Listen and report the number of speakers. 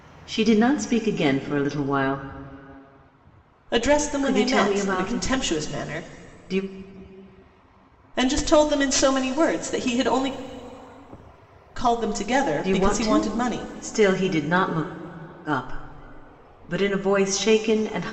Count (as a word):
two